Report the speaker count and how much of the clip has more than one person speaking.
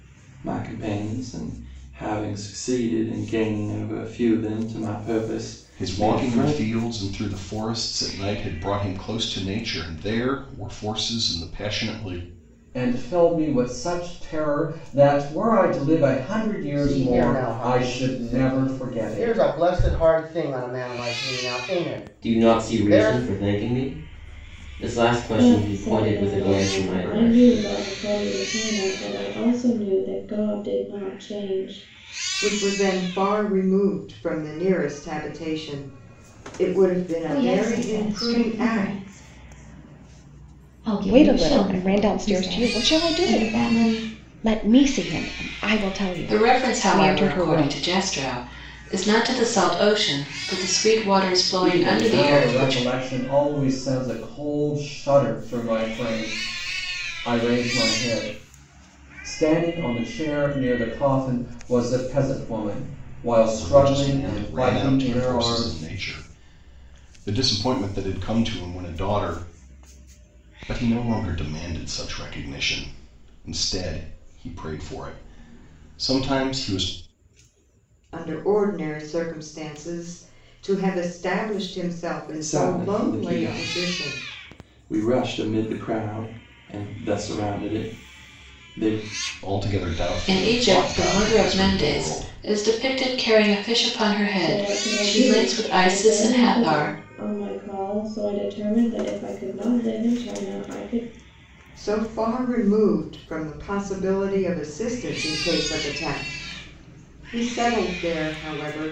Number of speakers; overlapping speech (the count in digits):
10, about 22%